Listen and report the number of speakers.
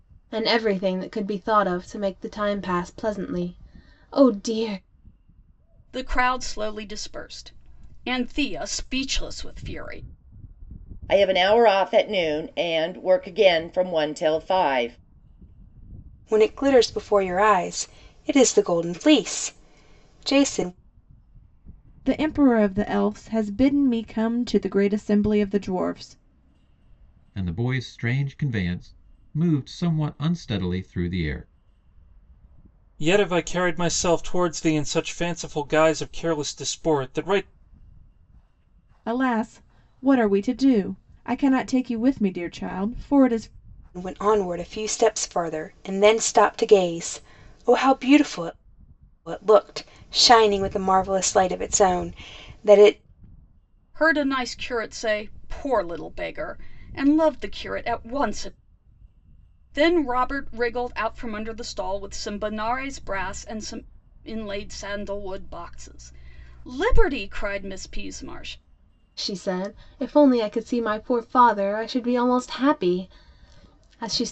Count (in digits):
7